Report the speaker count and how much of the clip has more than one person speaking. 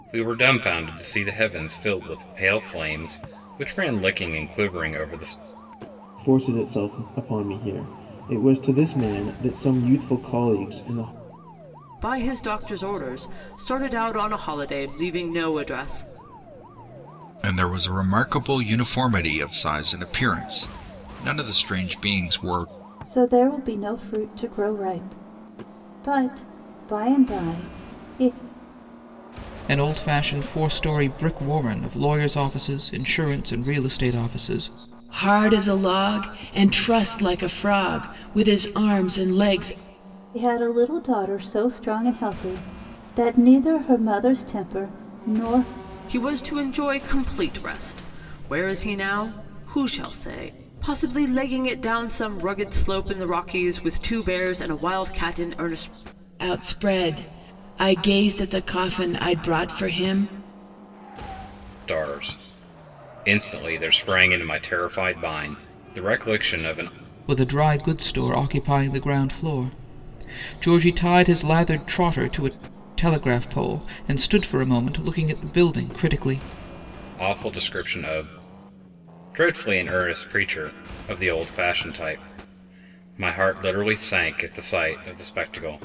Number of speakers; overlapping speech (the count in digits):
7, no overlap